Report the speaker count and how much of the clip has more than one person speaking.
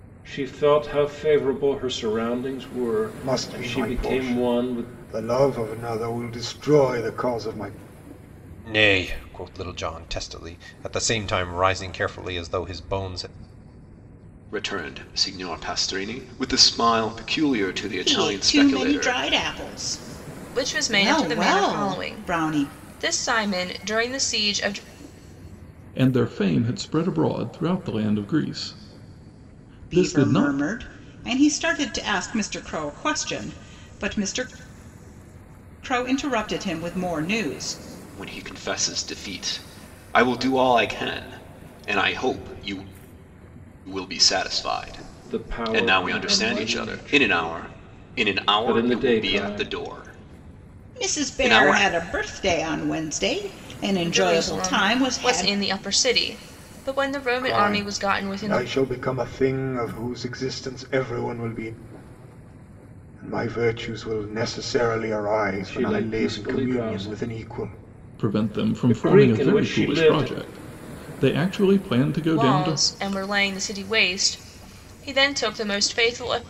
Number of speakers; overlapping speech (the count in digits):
7, about 25%